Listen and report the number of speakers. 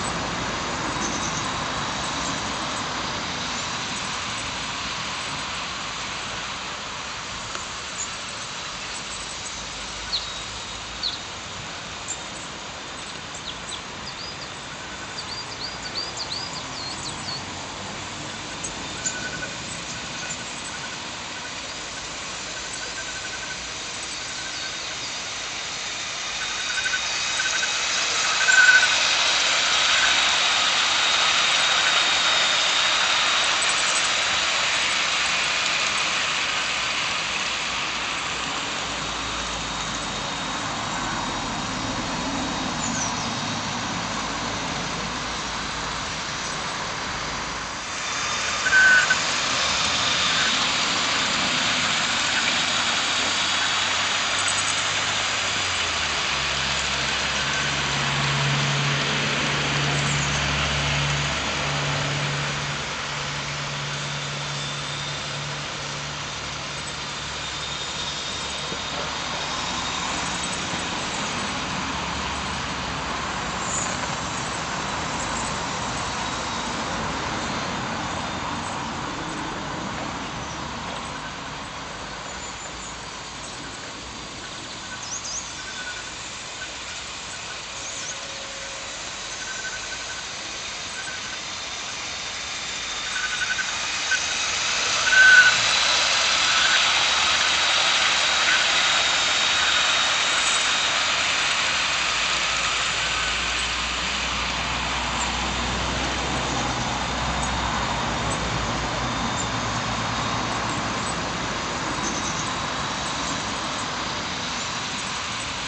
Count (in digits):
0